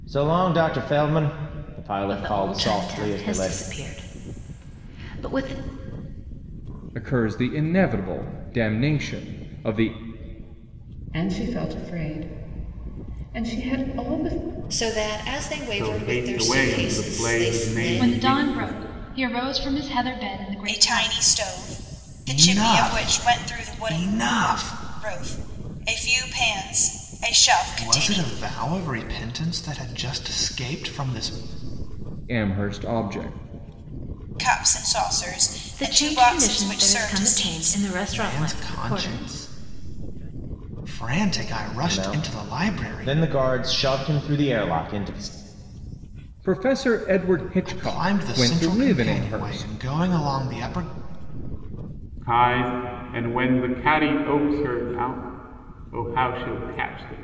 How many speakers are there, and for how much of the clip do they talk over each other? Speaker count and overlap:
9, about 25%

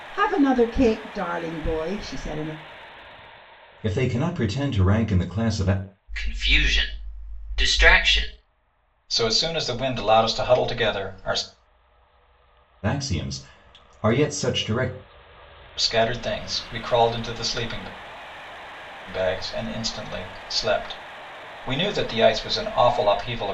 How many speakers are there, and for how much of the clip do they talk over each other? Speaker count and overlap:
4, no overlap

